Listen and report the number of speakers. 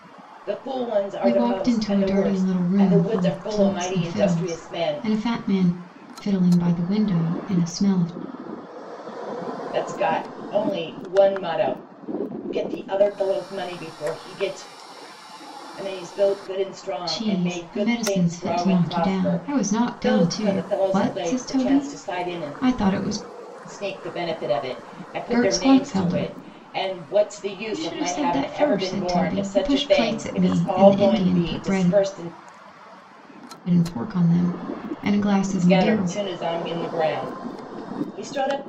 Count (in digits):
2